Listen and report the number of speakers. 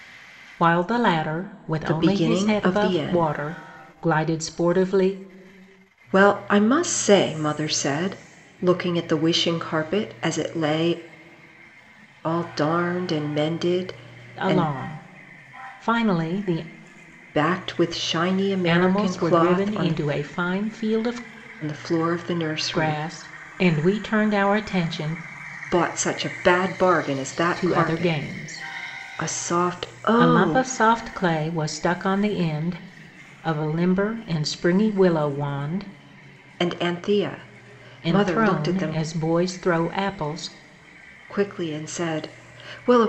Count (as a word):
two